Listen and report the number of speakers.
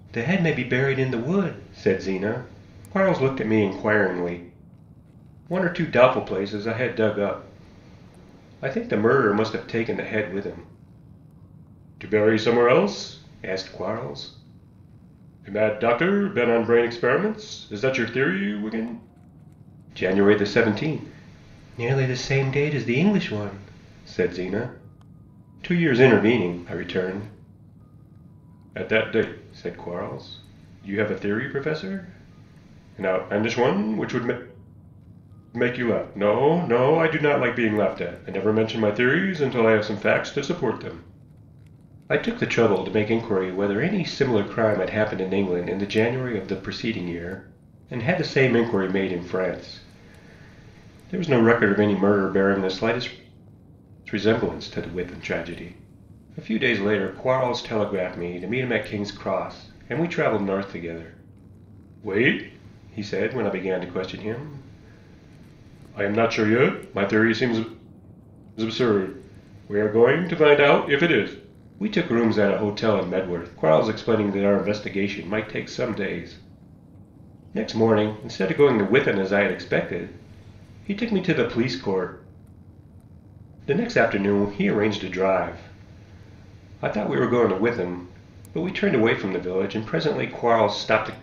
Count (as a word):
one